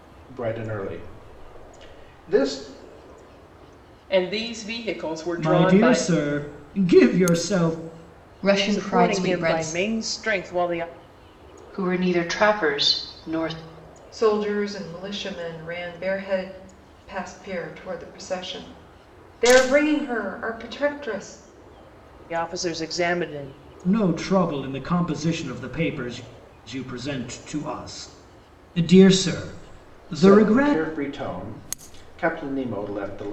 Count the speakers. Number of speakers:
seven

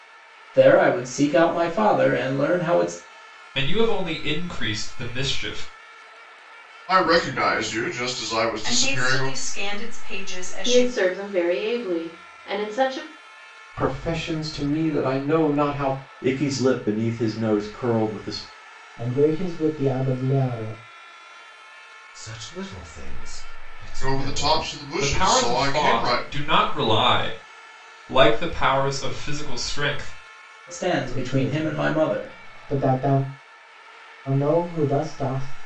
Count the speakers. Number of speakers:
nine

